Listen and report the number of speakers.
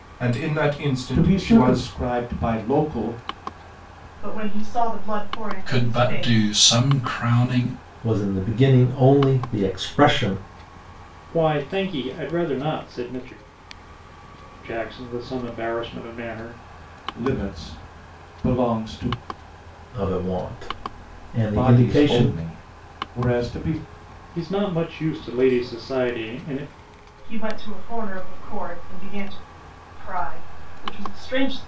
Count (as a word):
six